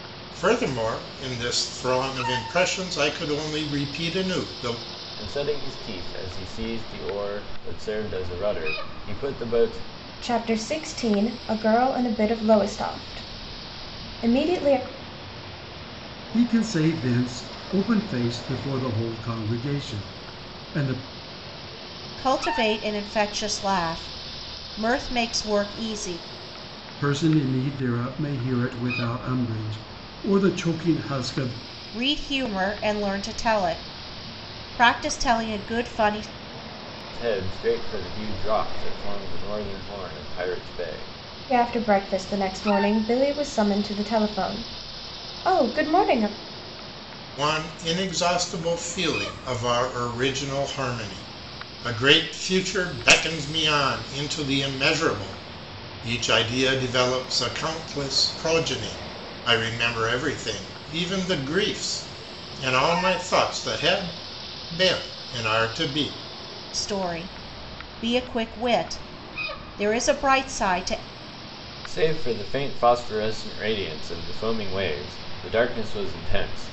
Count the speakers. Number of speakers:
5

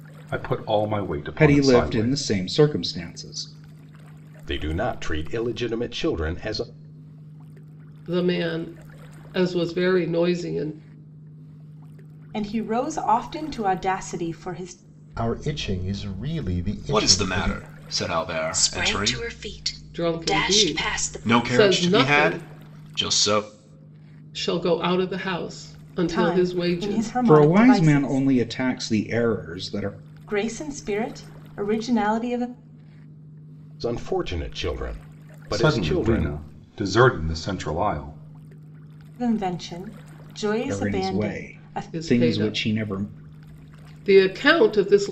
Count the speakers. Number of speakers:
8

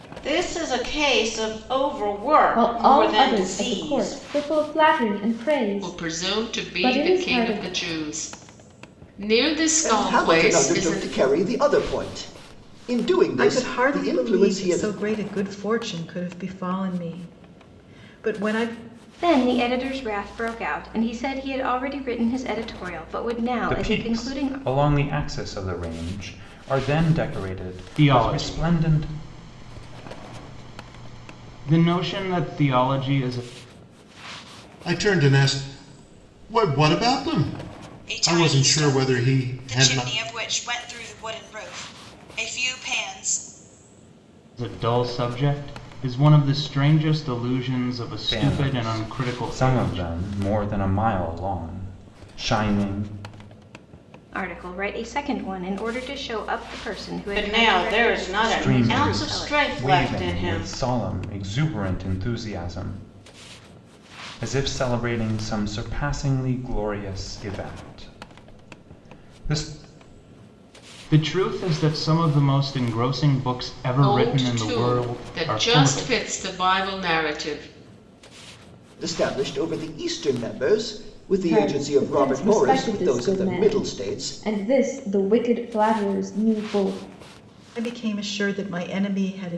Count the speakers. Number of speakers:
10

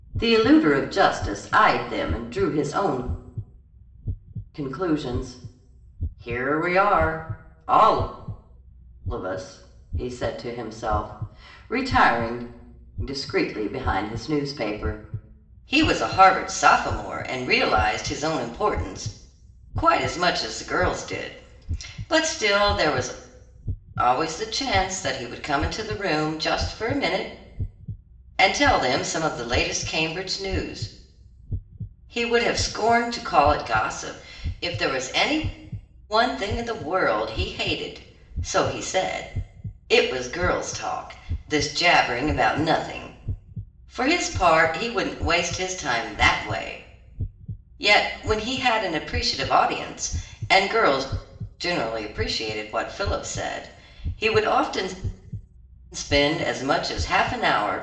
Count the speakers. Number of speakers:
1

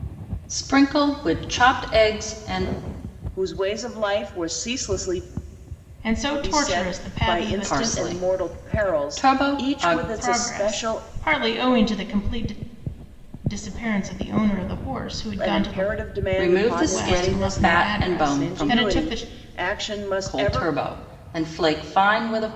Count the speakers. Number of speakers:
3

